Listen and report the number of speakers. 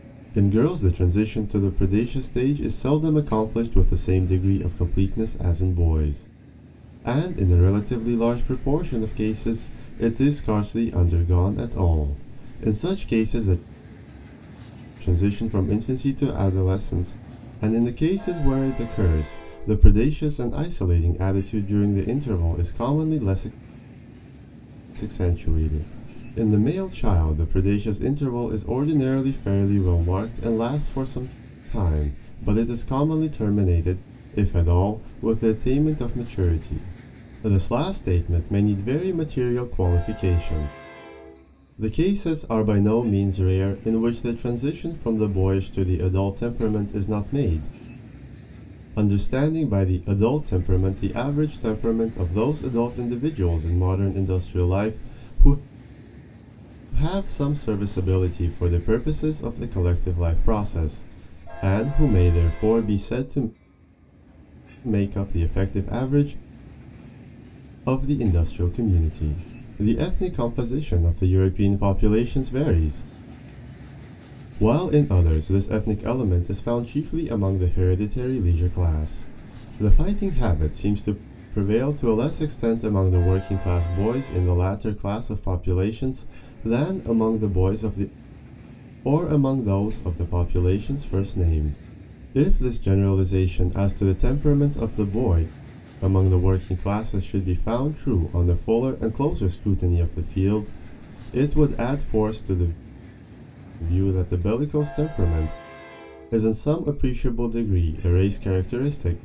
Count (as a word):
one